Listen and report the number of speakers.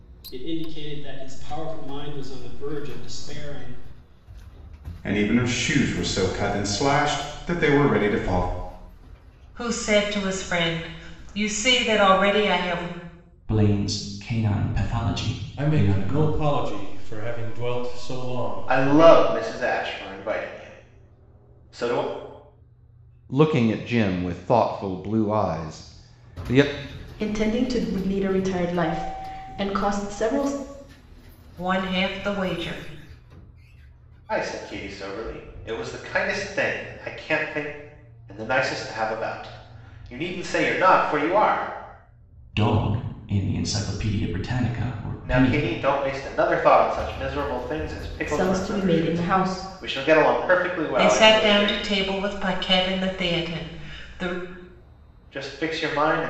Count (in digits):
8